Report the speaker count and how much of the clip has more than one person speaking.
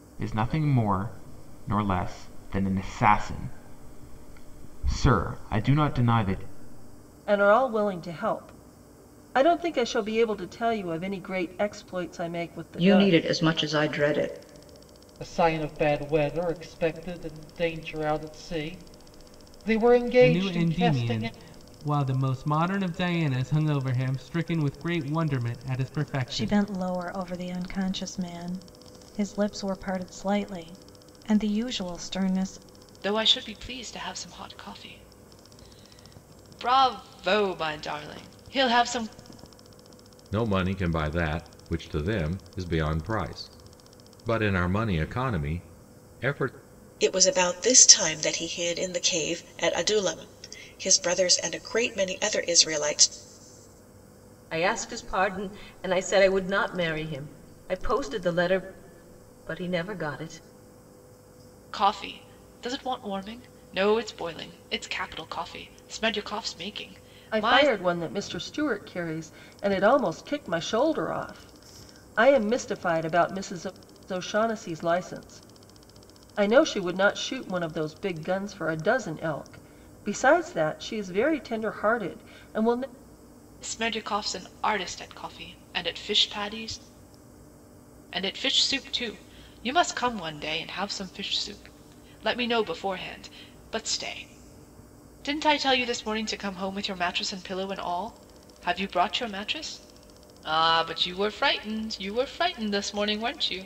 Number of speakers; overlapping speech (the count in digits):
10, about 2%